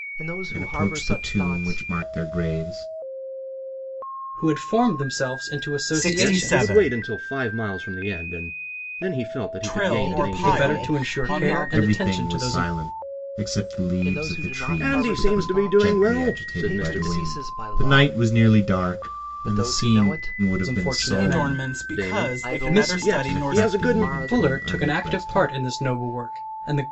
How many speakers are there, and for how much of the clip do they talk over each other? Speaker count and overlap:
5, about 57%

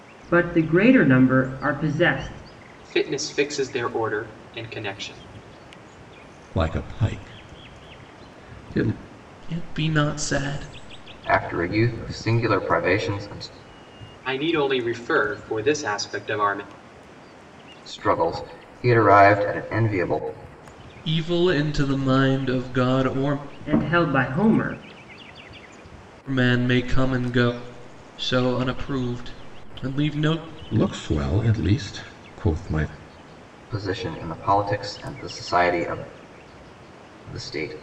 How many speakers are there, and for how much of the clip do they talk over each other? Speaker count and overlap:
5, no overlap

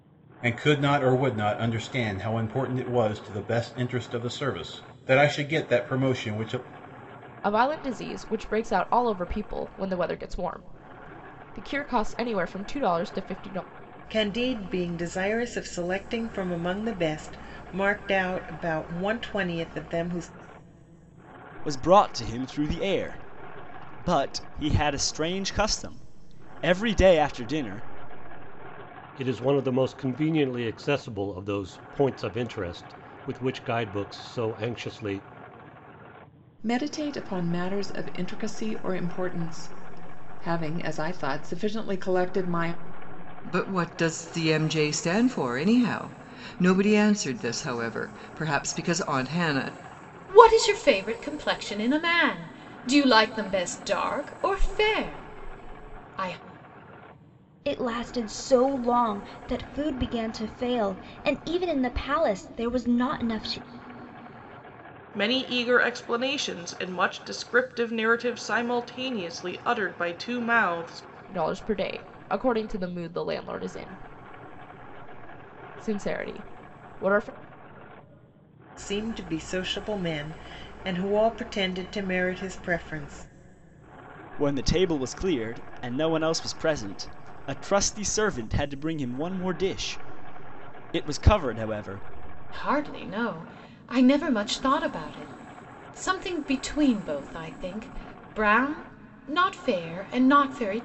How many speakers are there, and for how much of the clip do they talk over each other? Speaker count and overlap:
10, no overlap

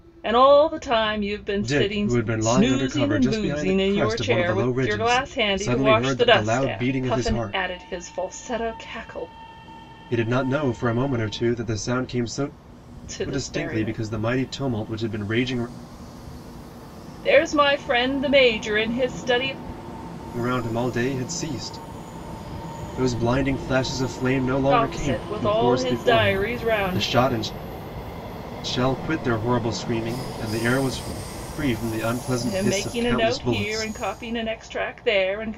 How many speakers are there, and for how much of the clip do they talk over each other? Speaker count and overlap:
2, about 32%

